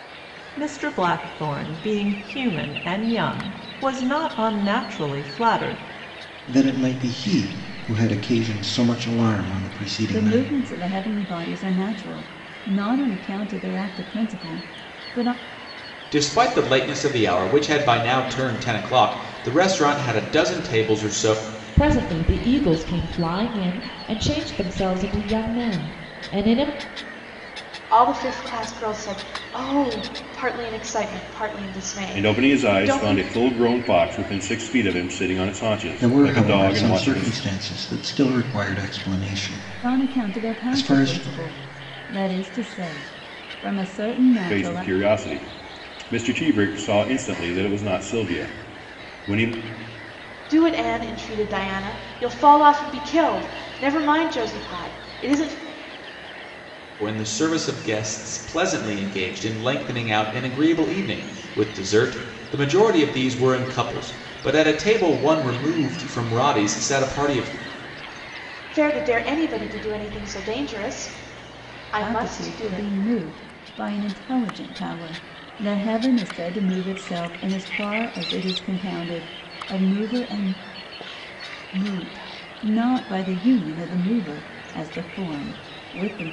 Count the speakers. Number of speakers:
seven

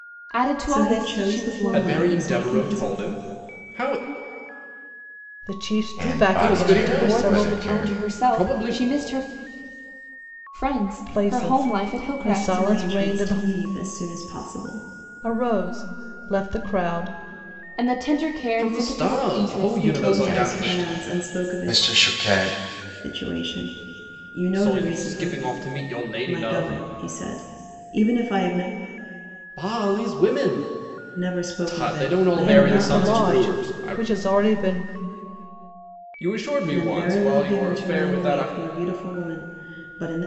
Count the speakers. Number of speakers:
five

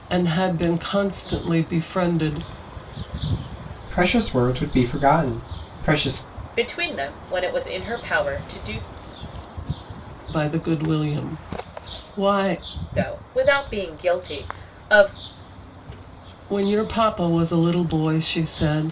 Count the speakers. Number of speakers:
three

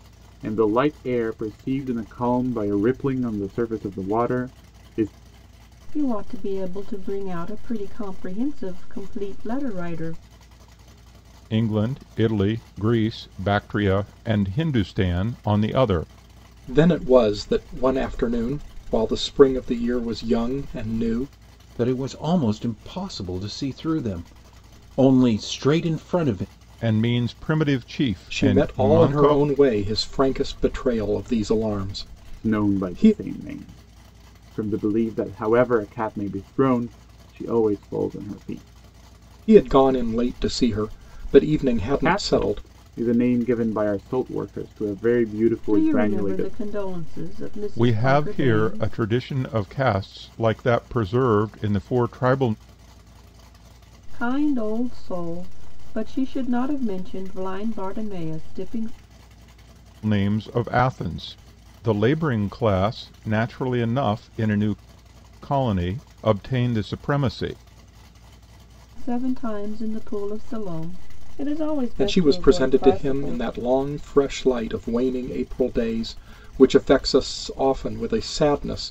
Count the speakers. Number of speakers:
five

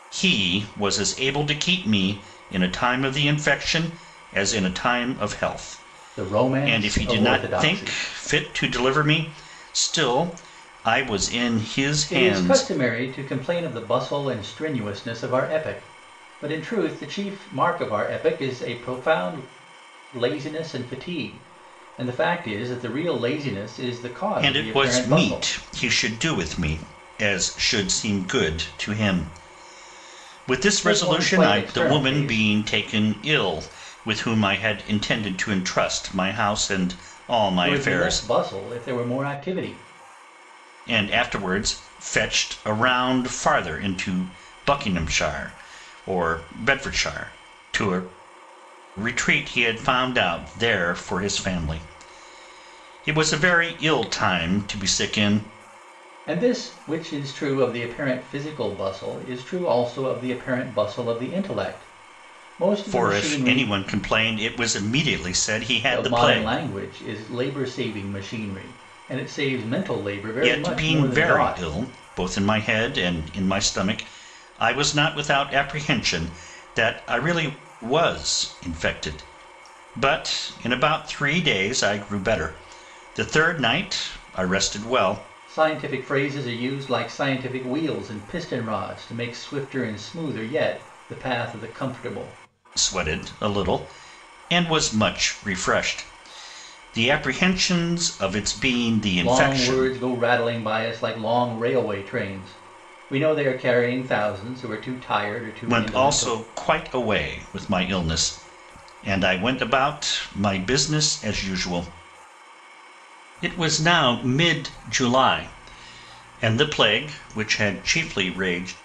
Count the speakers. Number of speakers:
two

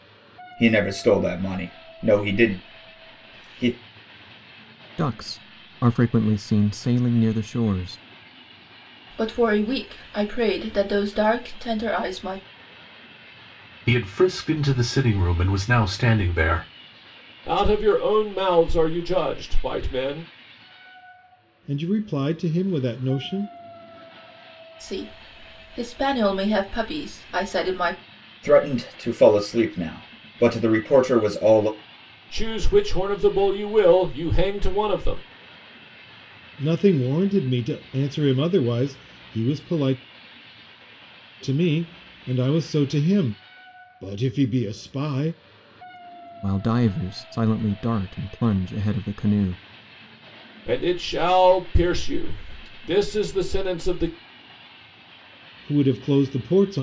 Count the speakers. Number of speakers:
six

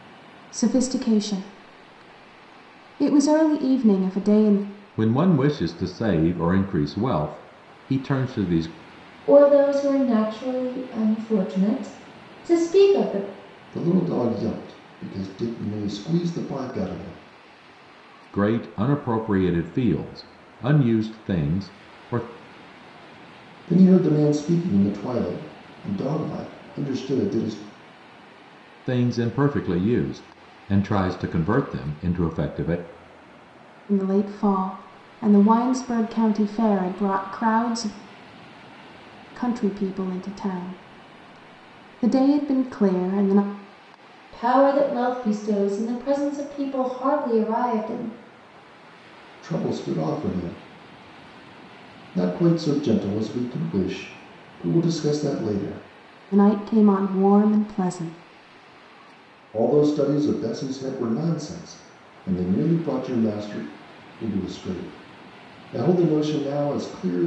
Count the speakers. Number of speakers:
four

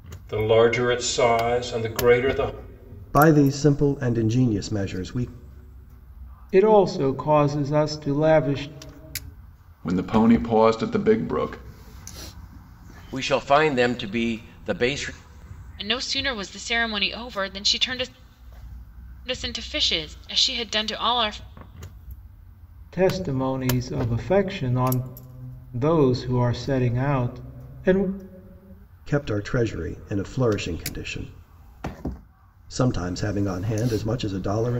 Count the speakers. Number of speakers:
six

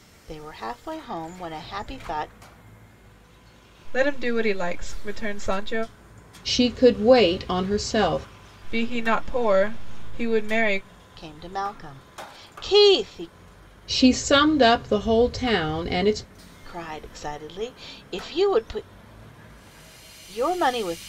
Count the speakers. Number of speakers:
three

